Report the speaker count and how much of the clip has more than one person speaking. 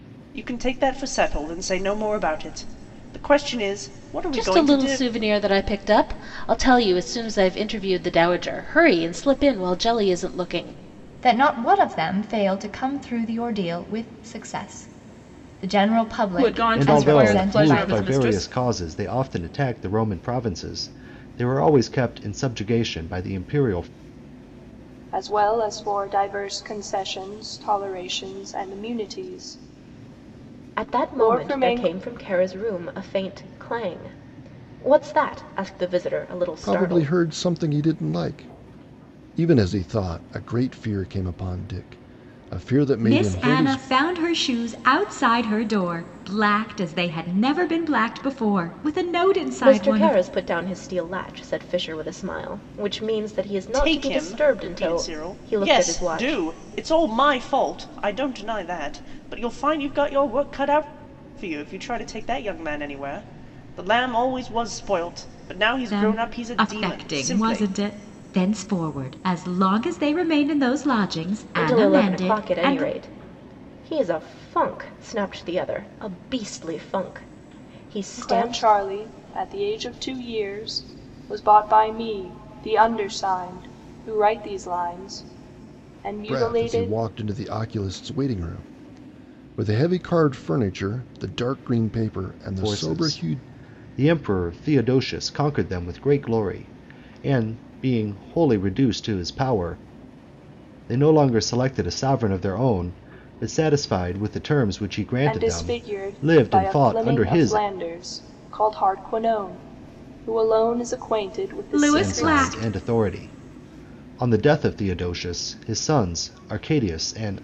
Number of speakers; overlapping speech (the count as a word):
nine, about 15%